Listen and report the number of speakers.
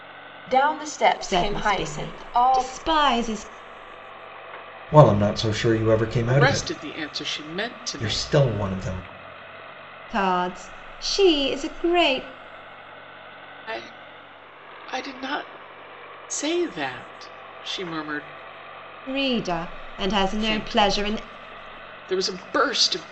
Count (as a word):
four